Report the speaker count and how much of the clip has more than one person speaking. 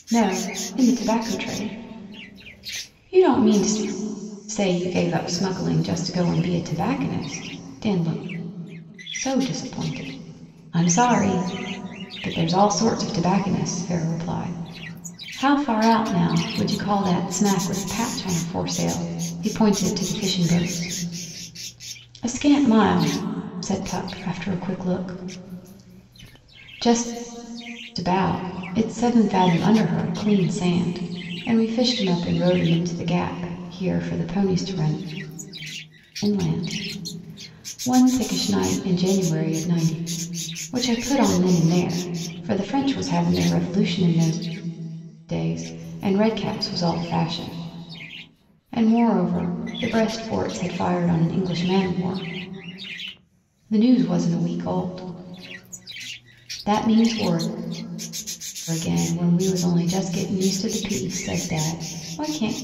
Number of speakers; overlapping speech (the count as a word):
one, no overlap